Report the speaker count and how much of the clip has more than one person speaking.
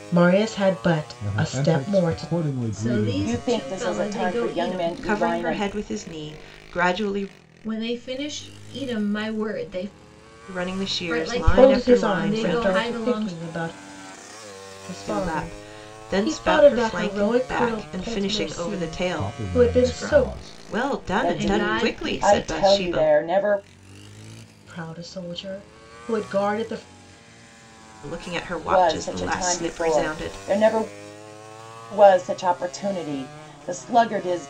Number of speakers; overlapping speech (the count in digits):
5, about 45%